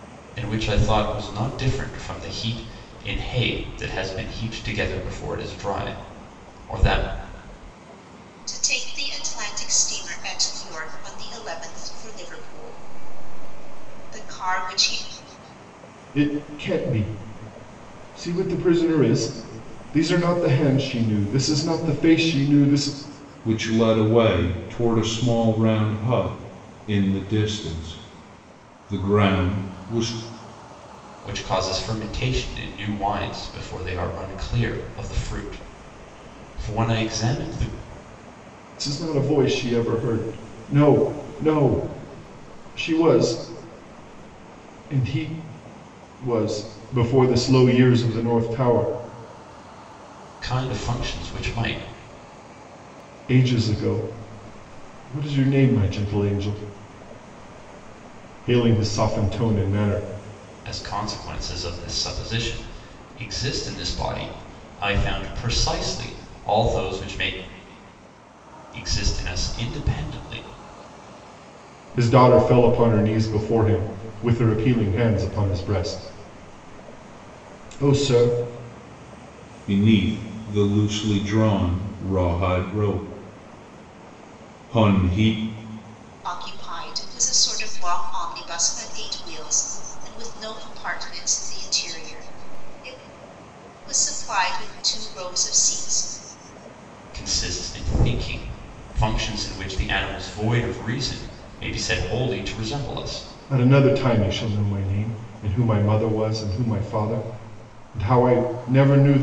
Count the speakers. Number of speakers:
four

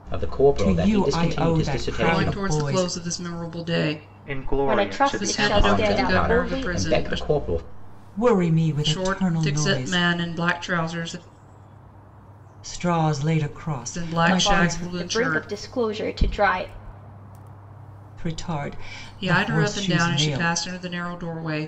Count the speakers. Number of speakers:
five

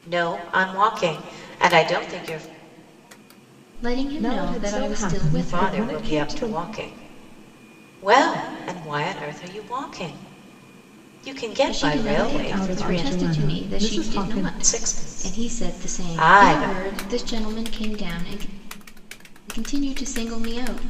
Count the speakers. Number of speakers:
three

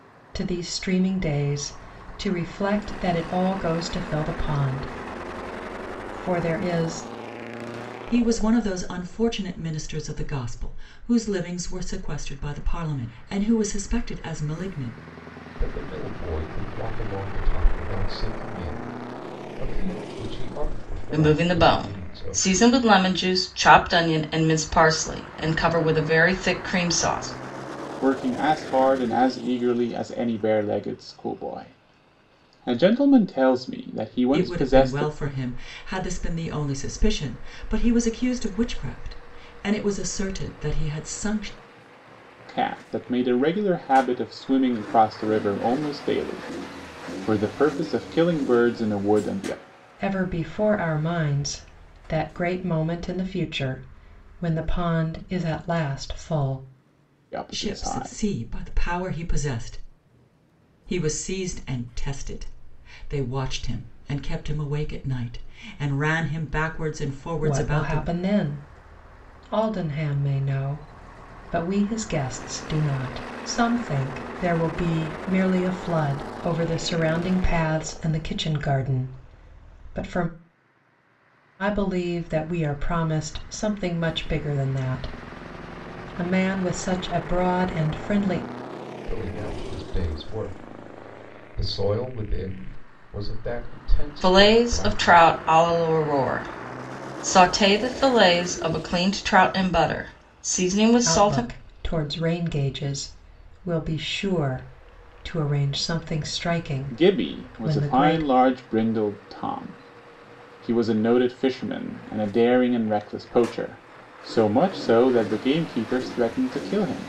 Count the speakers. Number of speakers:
five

